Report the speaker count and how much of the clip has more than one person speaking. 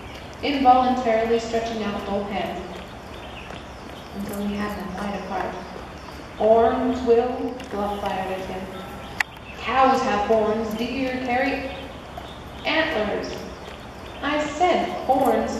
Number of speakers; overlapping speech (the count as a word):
one, no overlap